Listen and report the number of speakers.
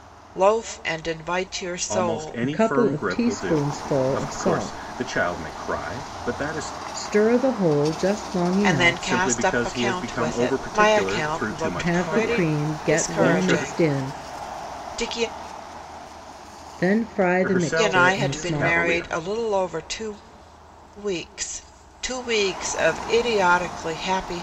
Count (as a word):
three